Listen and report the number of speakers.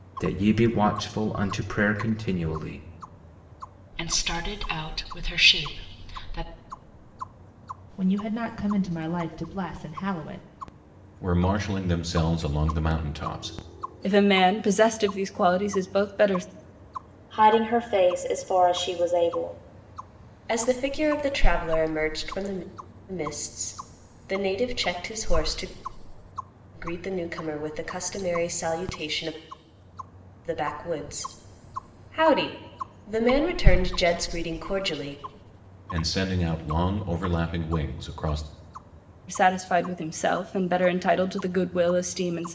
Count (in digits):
7